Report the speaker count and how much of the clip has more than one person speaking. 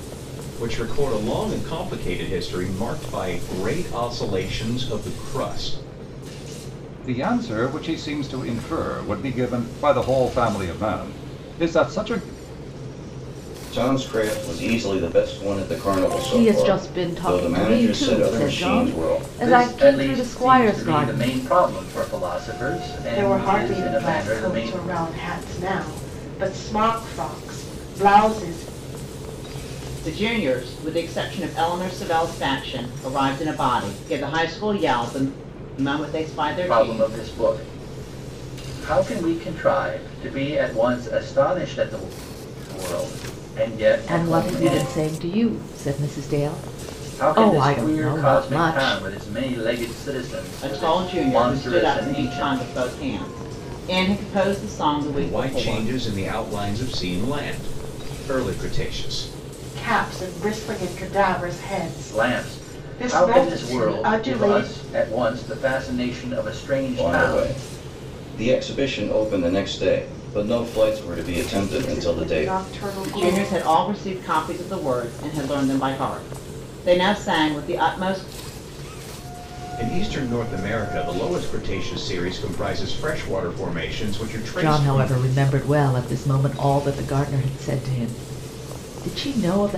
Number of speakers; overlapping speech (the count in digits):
7, about 20%